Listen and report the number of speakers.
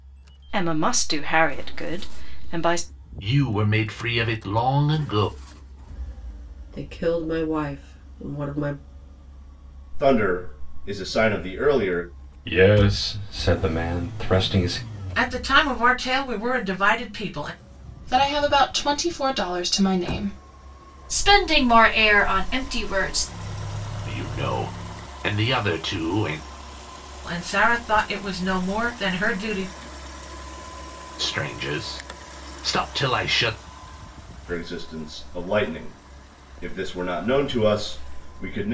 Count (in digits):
8